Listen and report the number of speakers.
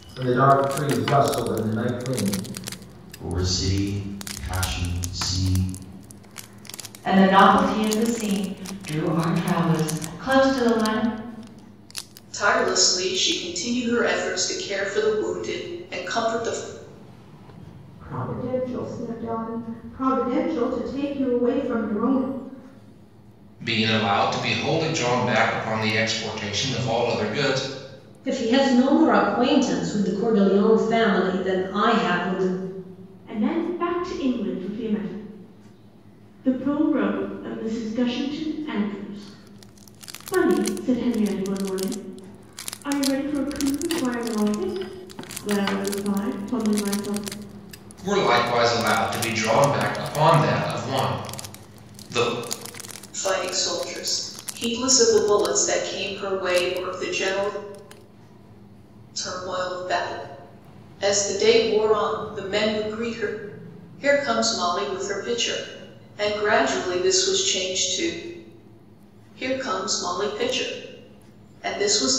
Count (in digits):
8